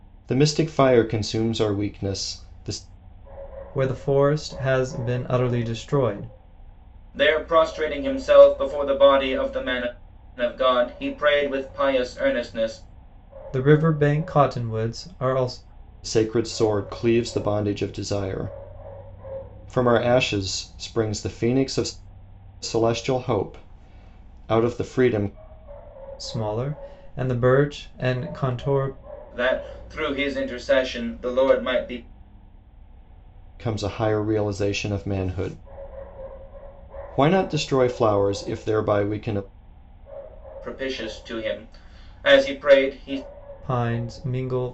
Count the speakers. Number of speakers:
3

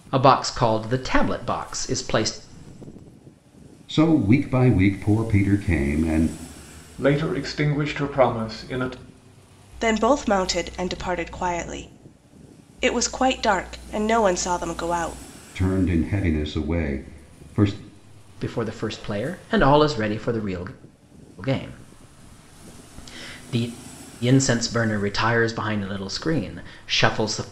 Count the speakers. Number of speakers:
4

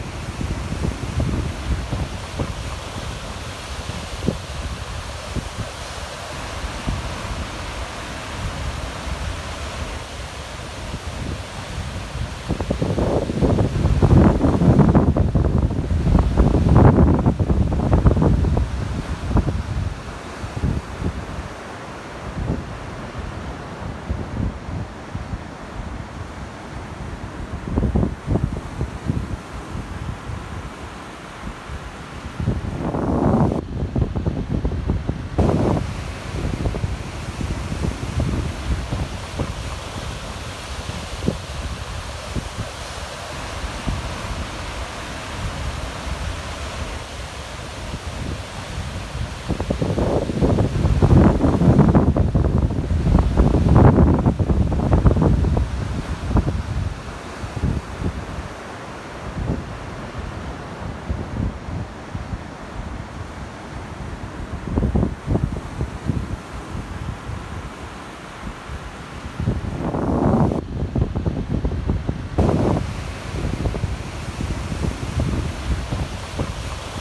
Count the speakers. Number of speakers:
0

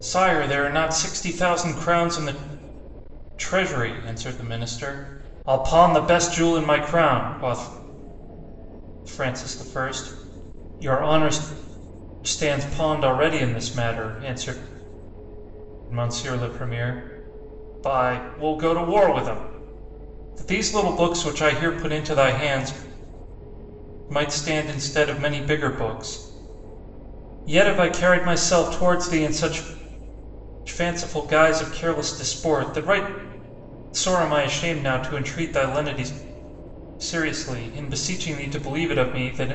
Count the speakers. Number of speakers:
1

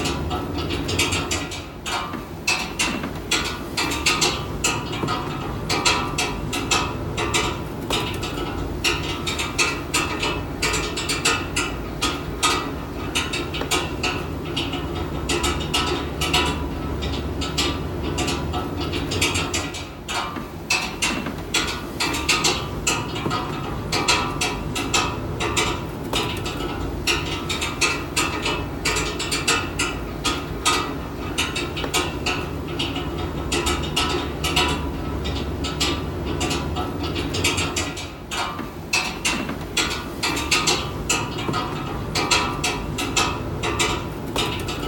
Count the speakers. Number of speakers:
0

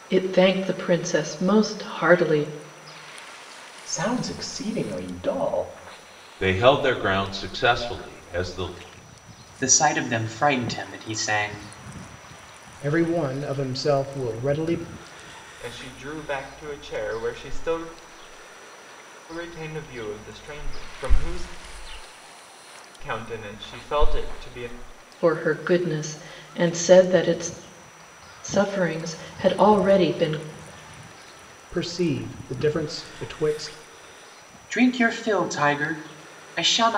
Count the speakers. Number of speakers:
6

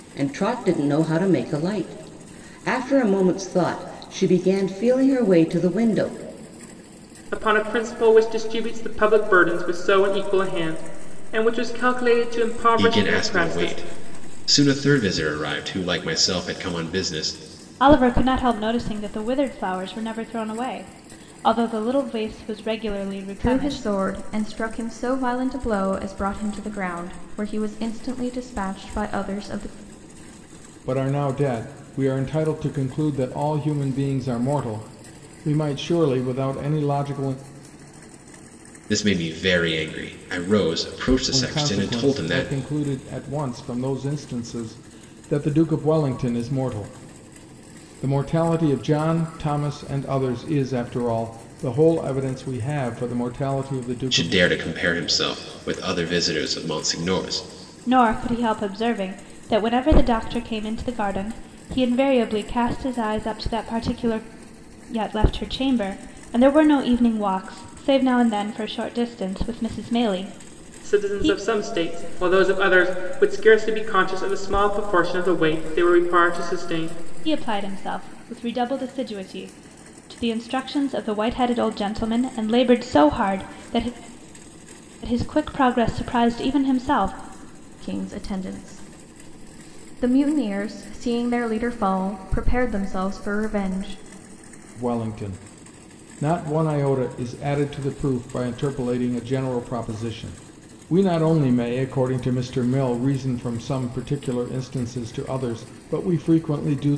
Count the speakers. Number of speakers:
6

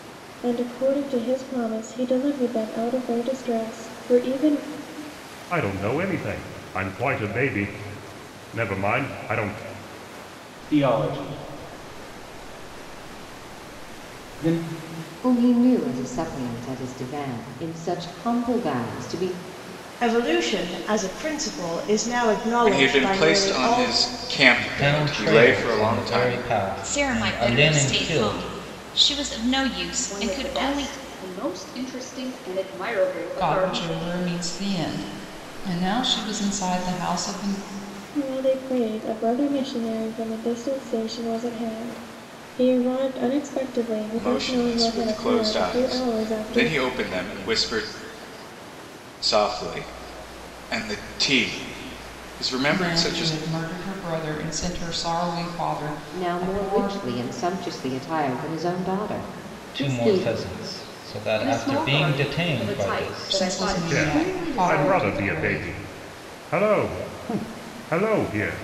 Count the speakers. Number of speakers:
10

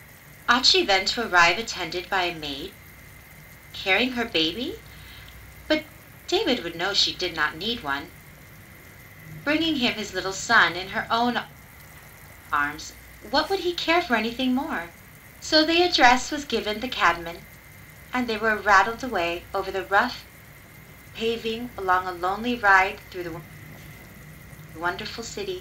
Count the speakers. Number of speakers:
1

